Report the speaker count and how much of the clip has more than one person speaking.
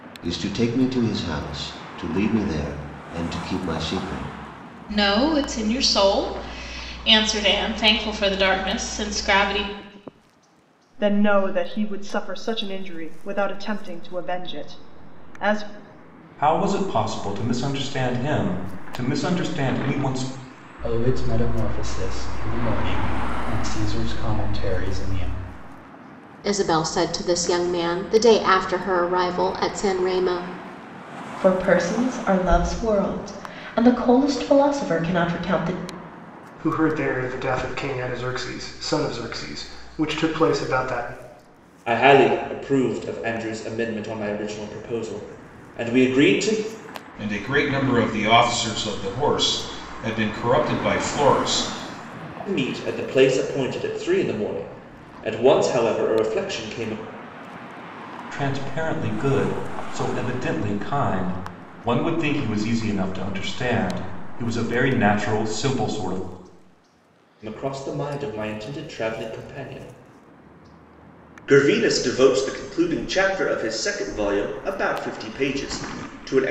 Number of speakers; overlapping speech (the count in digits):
10, no overlap